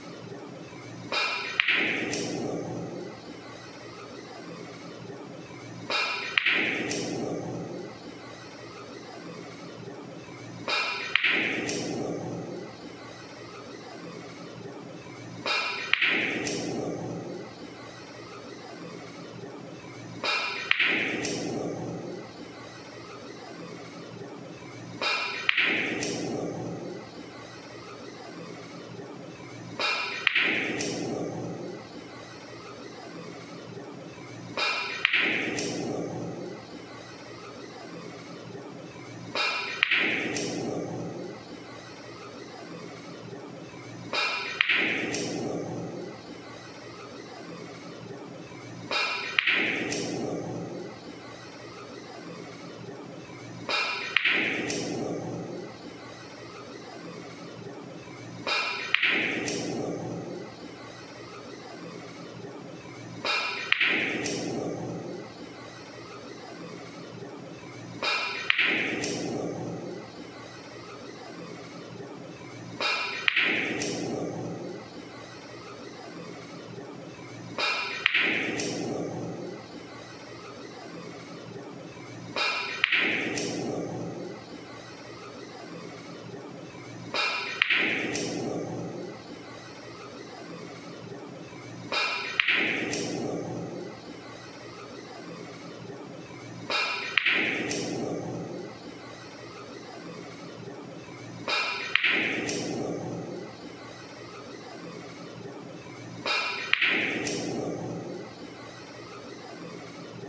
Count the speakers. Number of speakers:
0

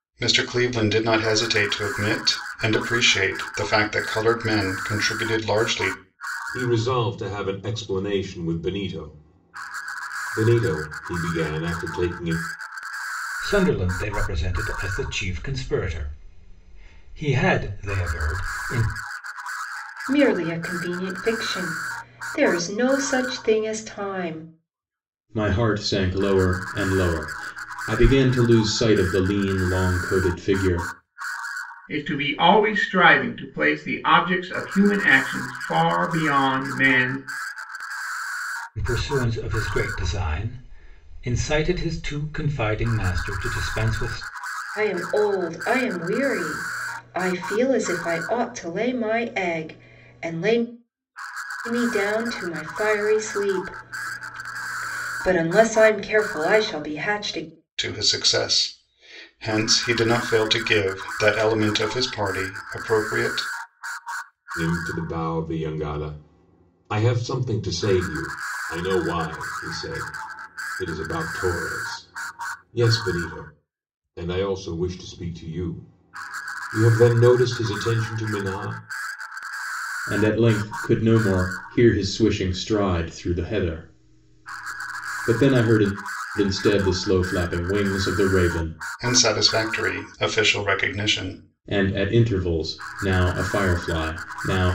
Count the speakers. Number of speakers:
6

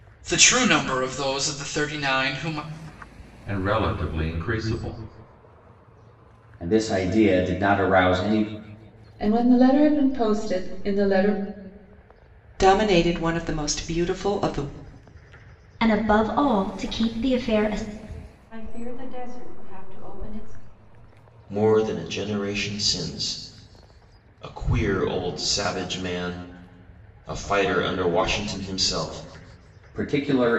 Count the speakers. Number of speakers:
8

